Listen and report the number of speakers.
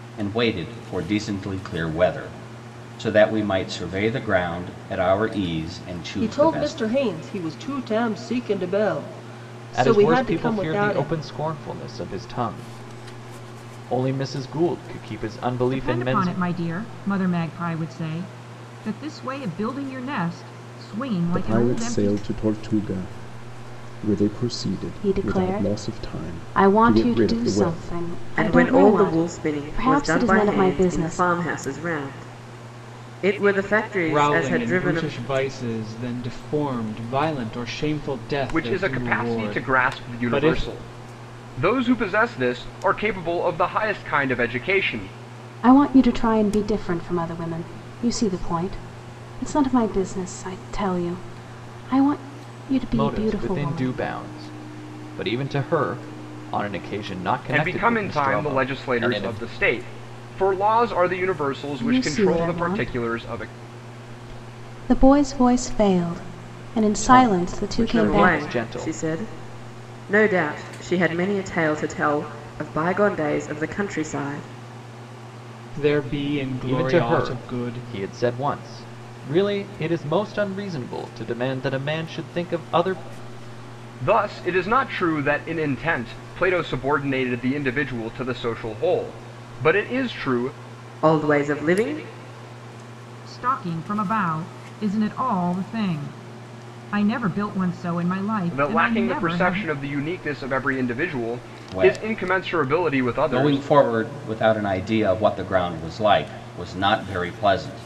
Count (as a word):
nine